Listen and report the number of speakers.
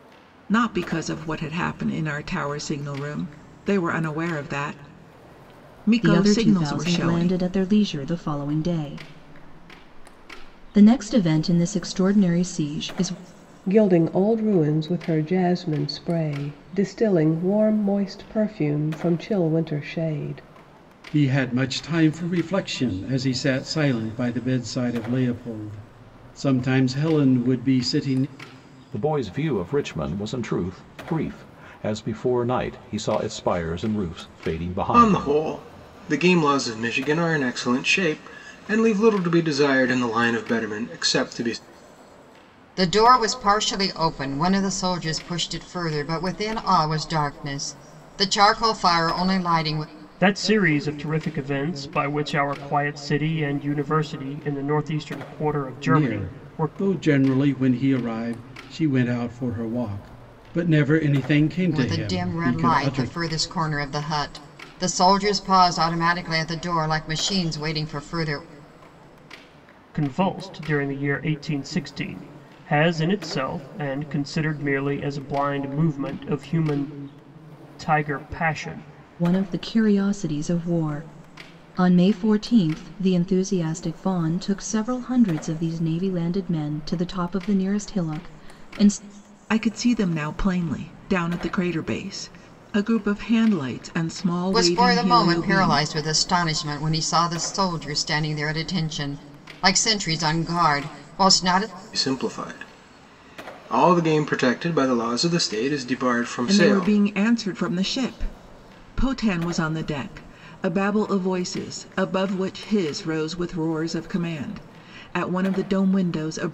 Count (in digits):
8